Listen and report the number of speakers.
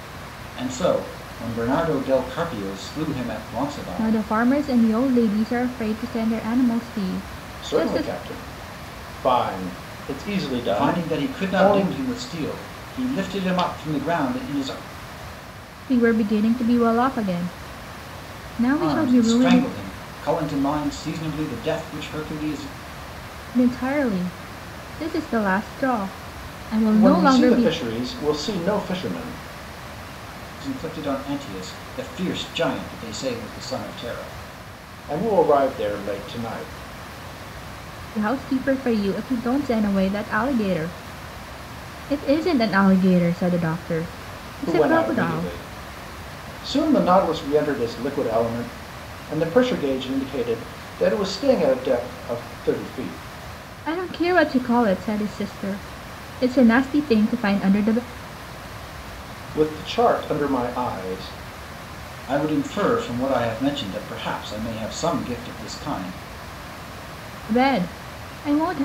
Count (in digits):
3